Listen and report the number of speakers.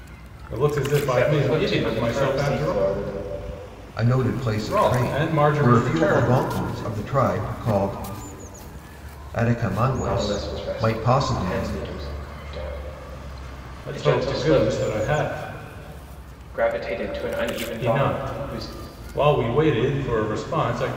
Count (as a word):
three